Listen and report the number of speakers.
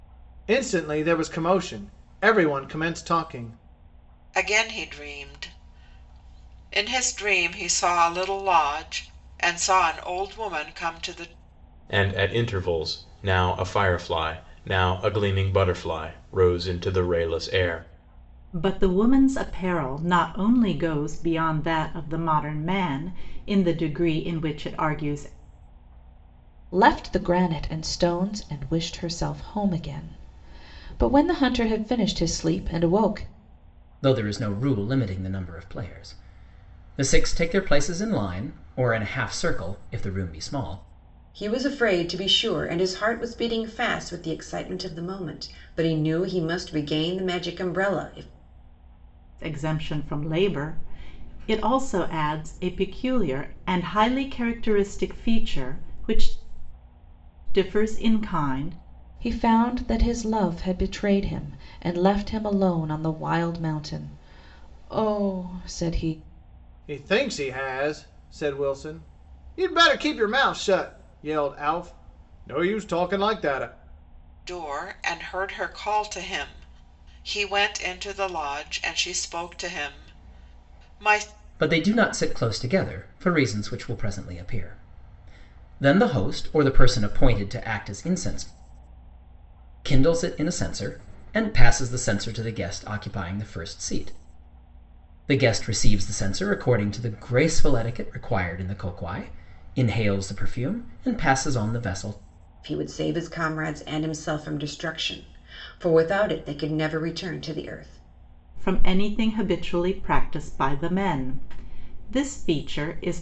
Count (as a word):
seven